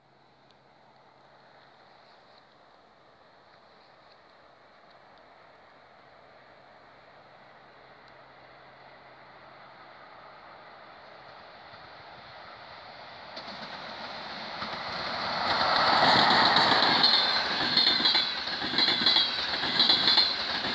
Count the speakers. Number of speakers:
0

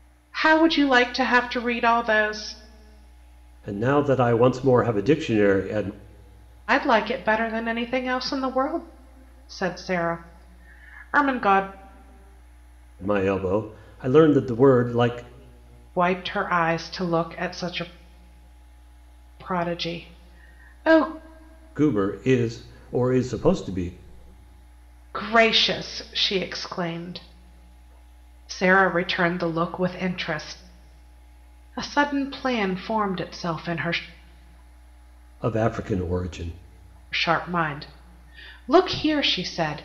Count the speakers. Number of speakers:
2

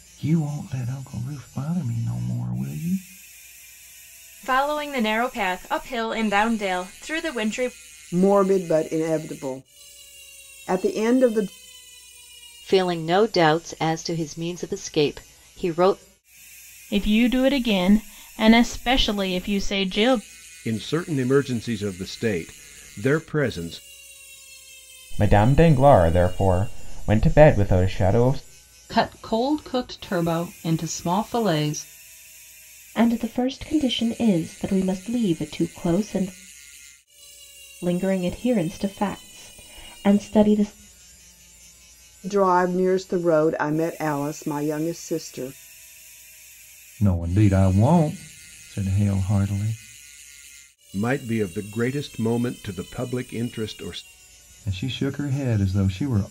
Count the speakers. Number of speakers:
9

